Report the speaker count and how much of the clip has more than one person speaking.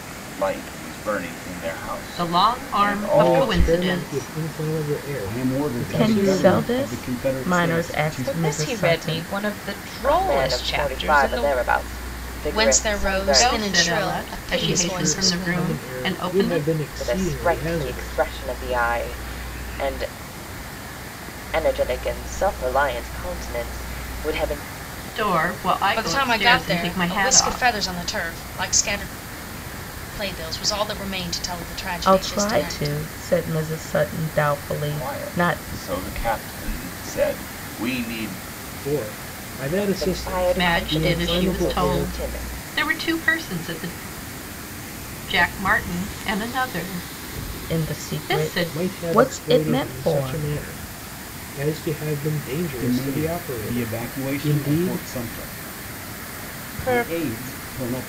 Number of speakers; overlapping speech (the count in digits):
8, about 43%